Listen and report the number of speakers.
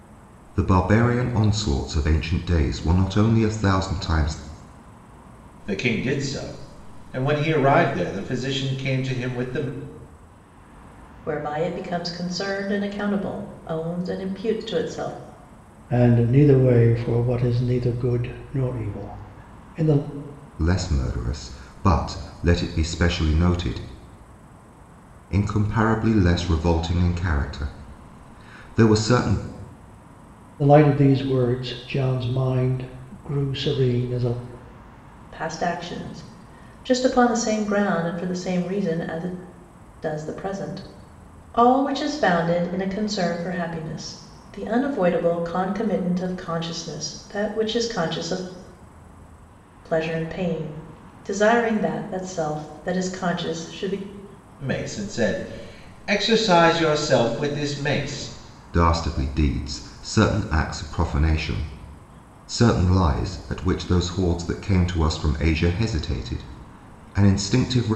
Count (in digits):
4